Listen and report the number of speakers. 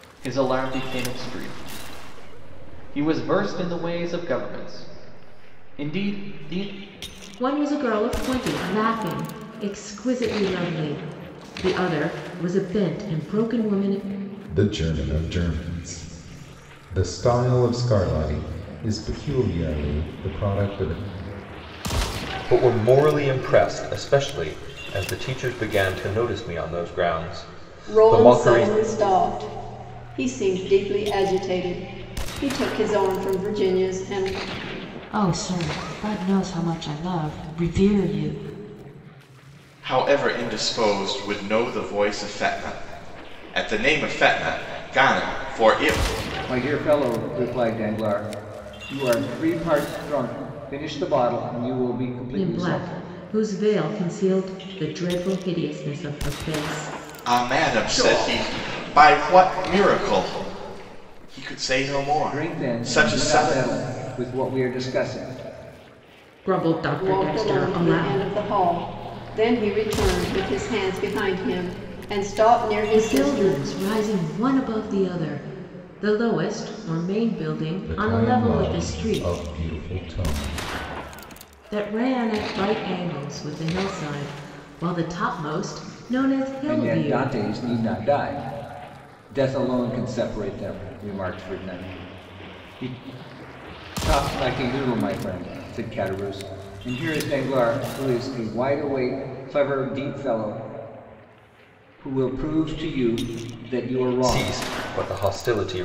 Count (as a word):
eight